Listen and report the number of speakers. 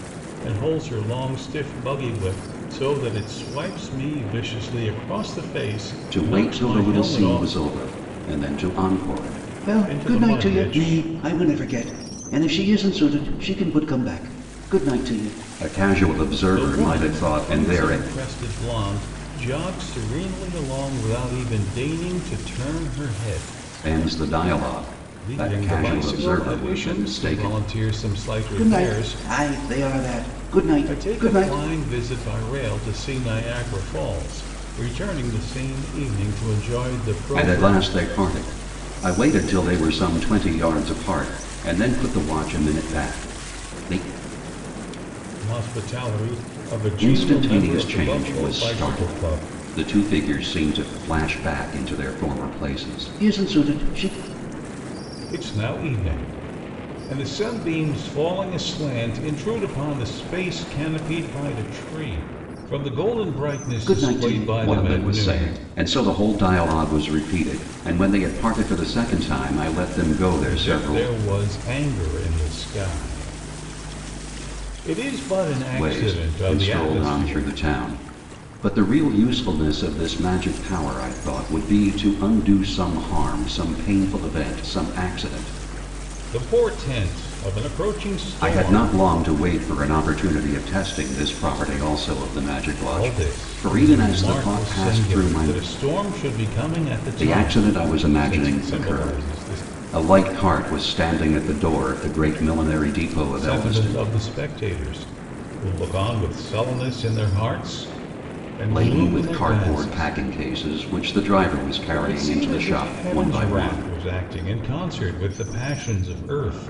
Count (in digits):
2